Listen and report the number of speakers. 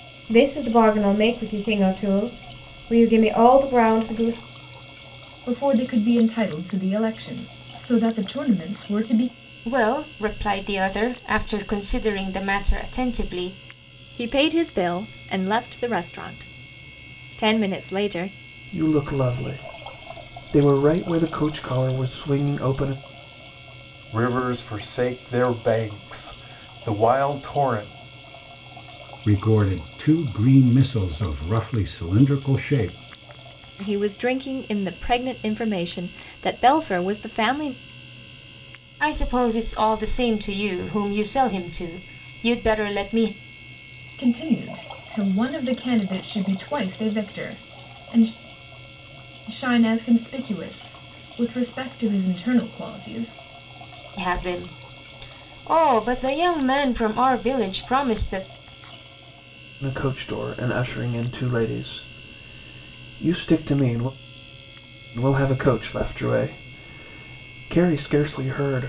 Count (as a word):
seven